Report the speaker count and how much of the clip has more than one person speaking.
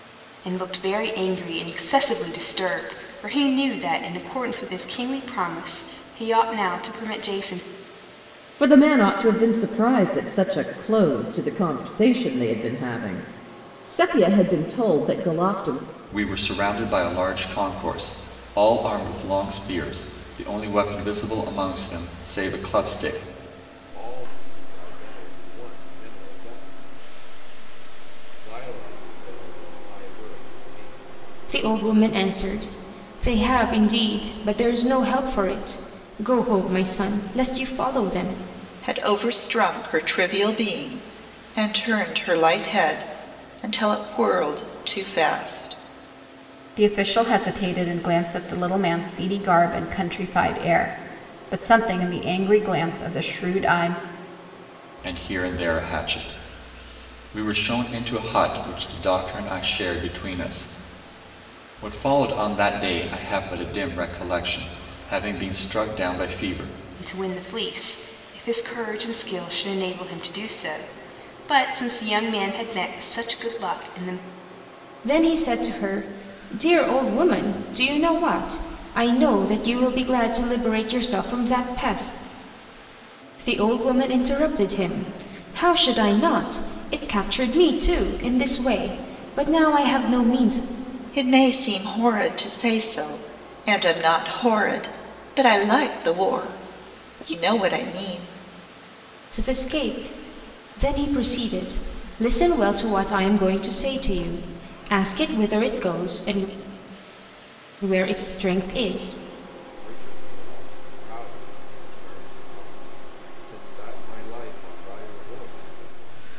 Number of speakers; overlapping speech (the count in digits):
7, no overlap